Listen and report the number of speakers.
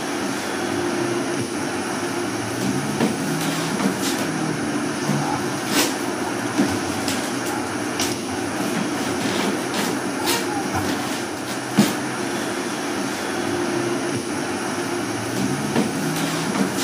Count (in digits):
0